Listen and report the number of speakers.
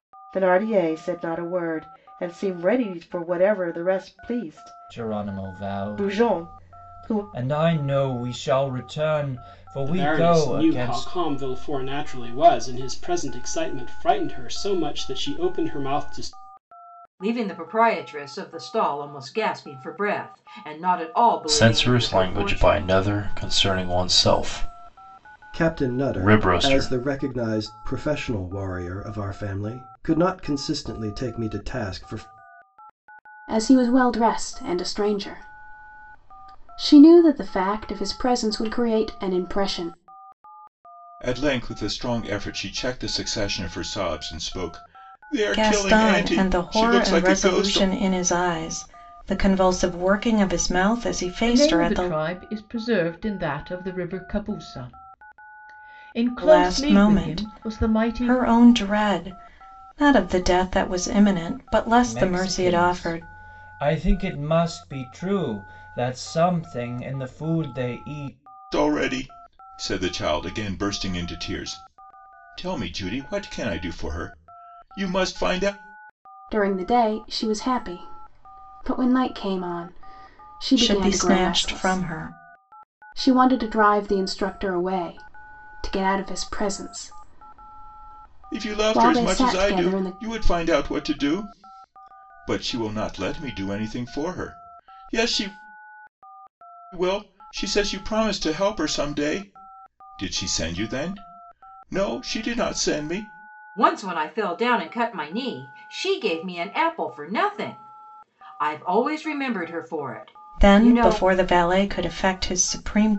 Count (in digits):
10